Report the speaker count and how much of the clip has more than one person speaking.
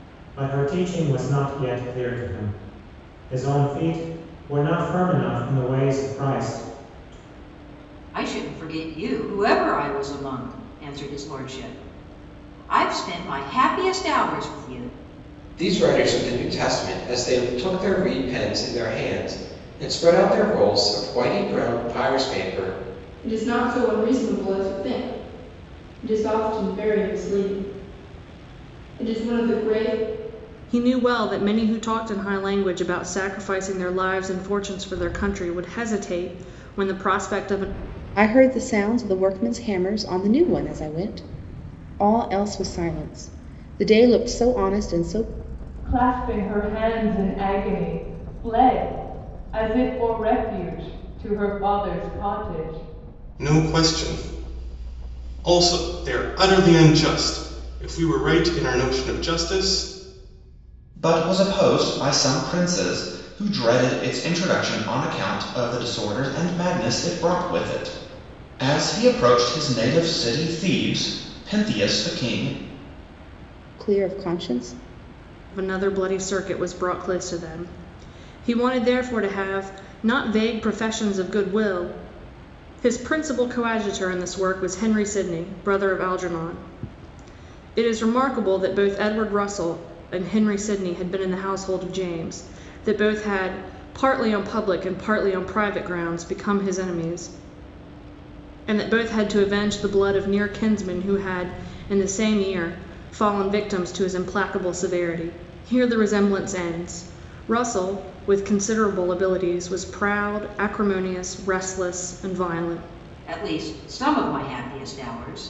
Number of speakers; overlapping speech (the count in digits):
9, no overlap